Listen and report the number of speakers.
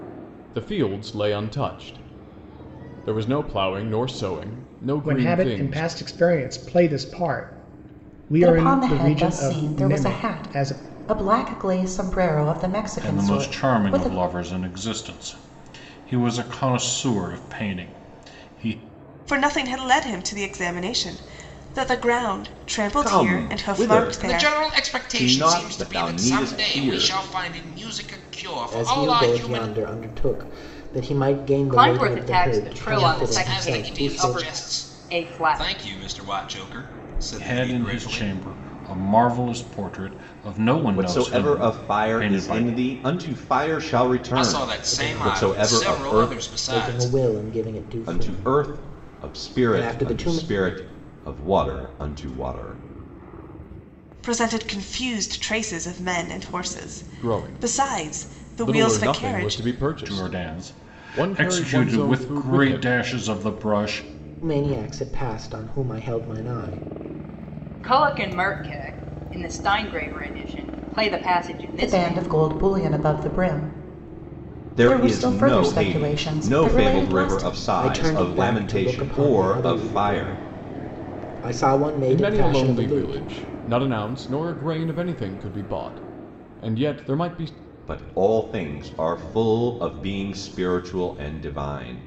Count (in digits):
9